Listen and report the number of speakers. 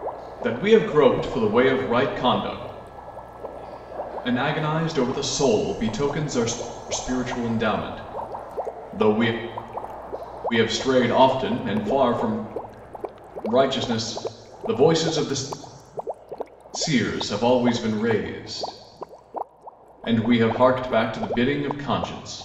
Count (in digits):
1